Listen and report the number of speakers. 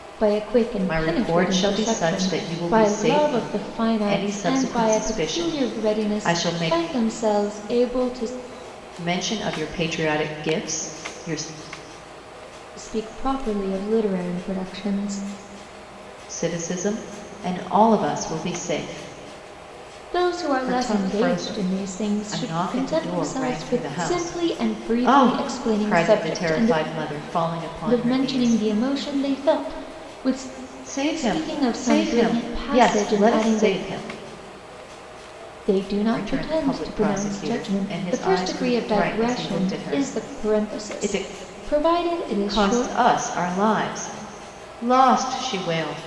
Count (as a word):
two